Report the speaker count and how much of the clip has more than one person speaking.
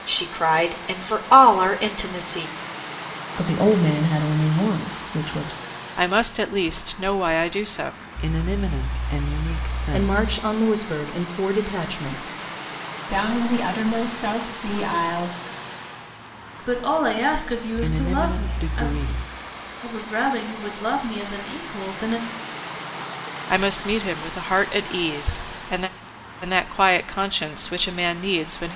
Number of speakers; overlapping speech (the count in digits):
7, about 6%